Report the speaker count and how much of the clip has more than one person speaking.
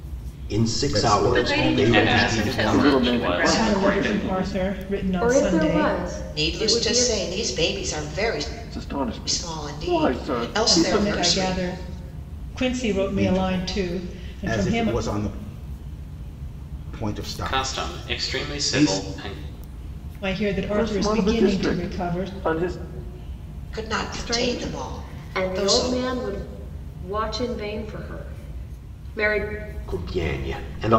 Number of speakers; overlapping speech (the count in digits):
8, about 47%